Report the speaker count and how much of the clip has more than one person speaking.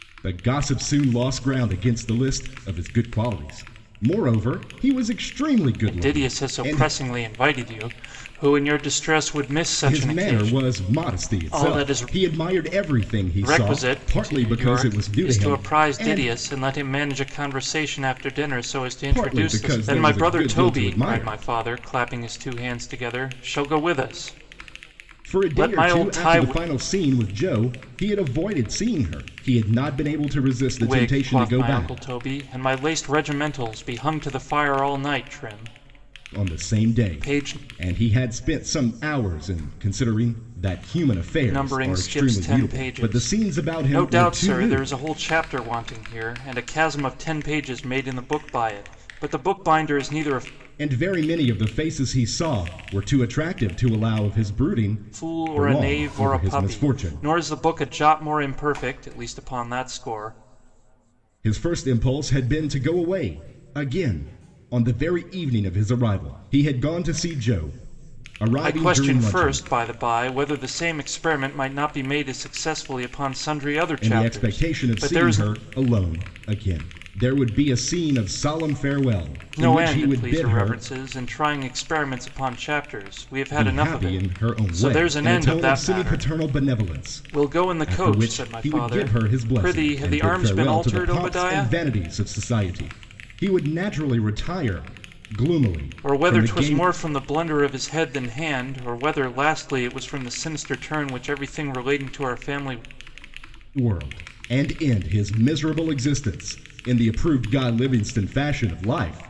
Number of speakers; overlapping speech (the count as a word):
two, about 27%